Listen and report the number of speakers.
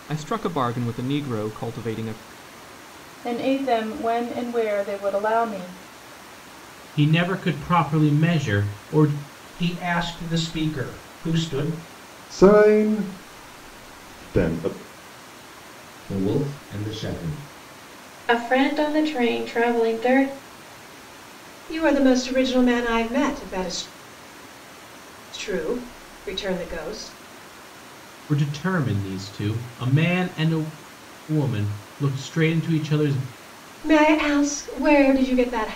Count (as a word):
eight